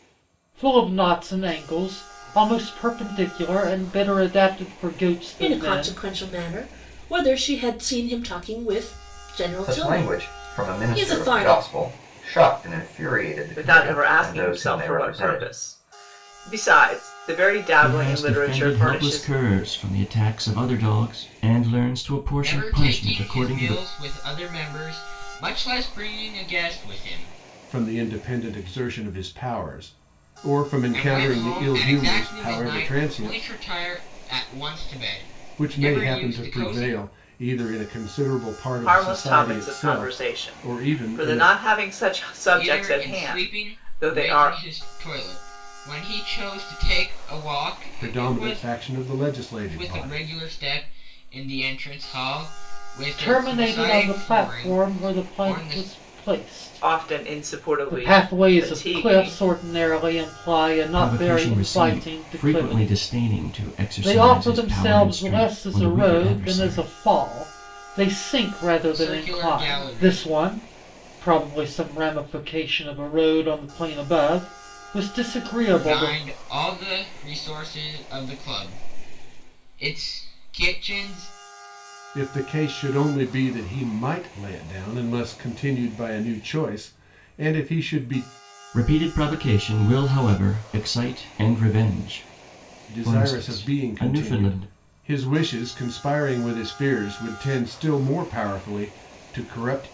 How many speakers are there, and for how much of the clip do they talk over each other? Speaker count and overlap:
7, about 32%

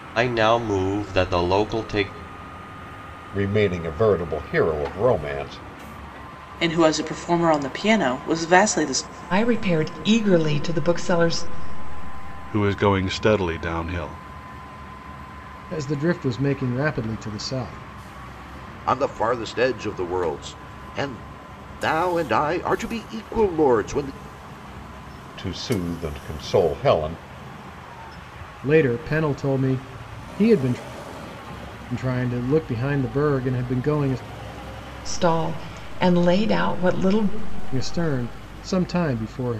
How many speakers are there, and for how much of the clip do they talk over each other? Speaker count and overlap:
7, no overlap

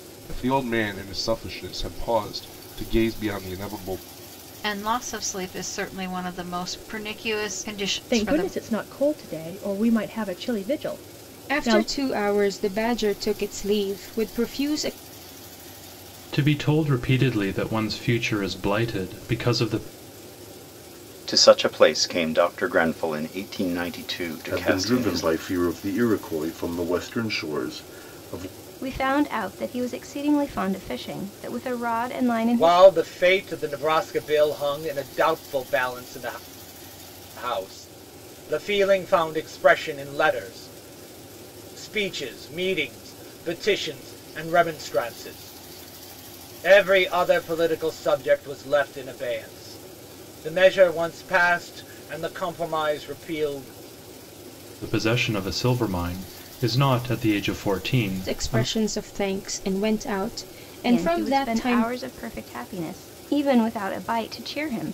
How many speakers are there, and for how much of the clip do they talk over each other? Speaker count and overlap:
9, about 6%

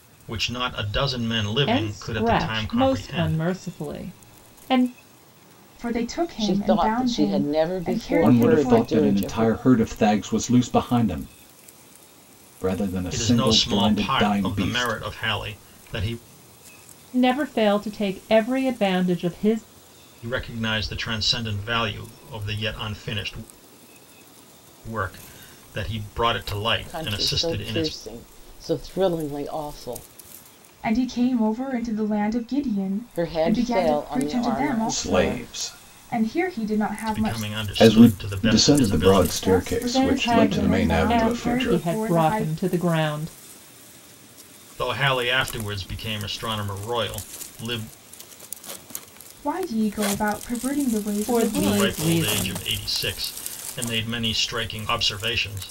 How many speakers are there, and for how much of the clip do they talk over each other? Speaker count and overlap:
5, about 34%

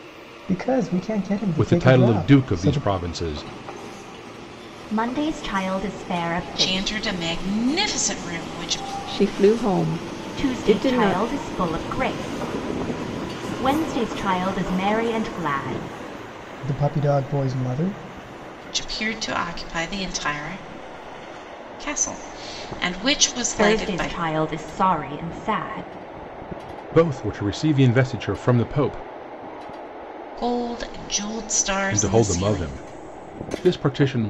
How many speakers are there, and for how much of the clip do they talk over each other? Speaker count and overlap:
5, about 13%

